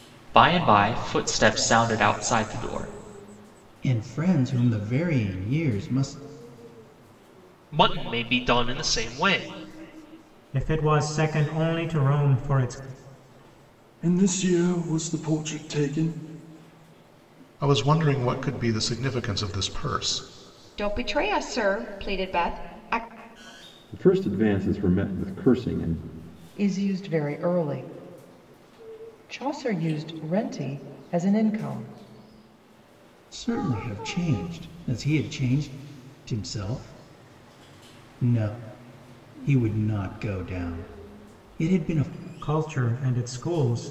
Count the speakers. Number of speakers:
9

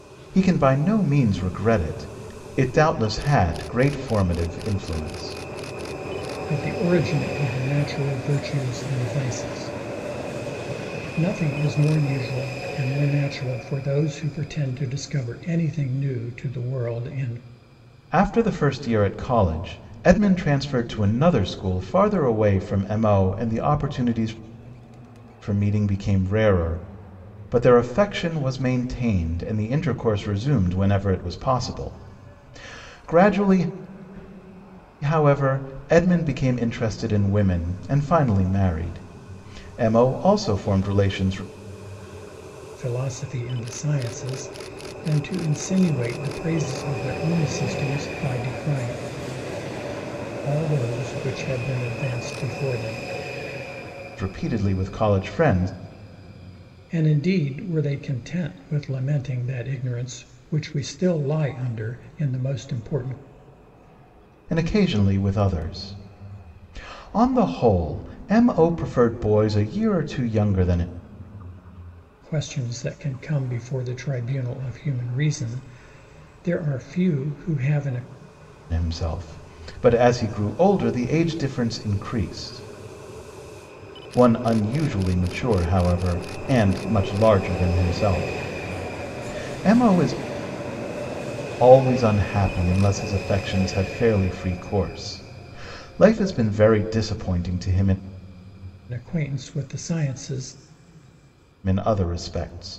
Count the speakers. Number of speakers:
2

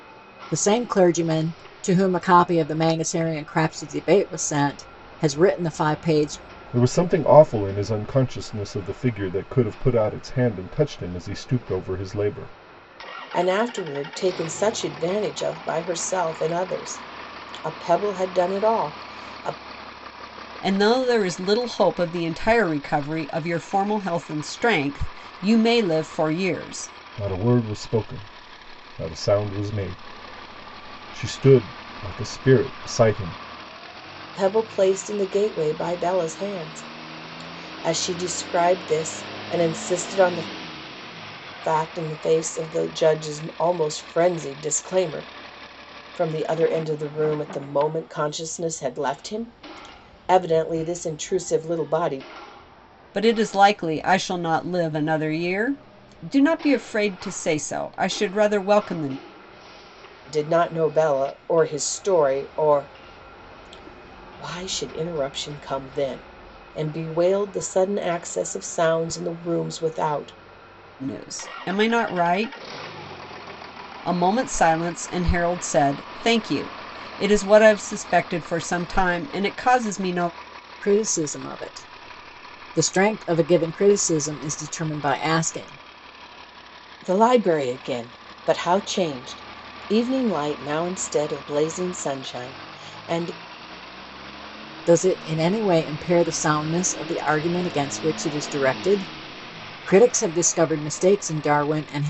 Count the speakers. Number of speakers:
4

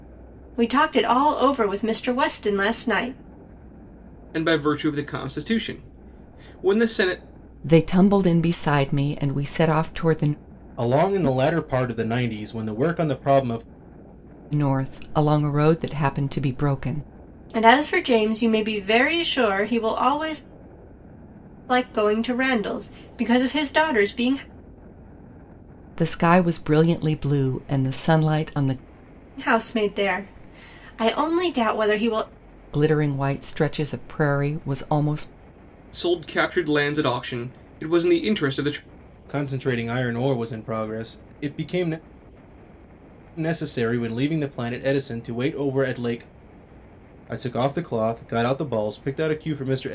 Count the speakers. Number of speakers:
4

